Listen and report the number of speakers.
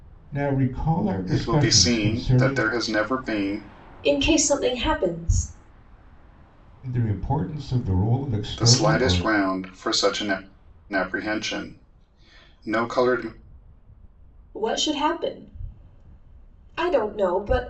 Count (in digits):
3